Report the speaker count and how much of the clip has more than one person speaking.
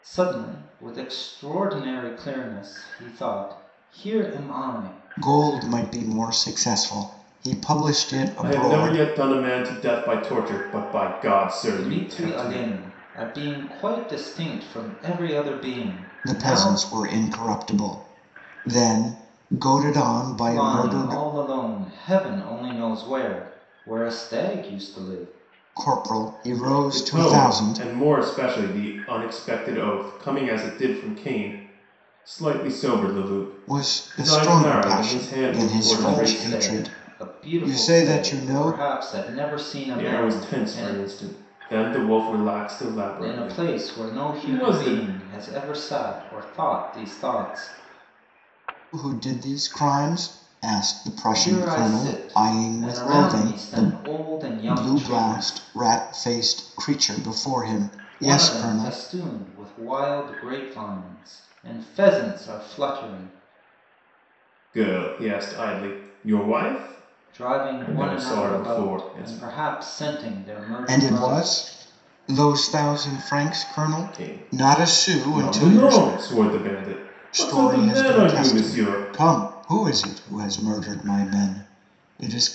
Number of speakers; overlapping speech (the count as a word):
three, about 28%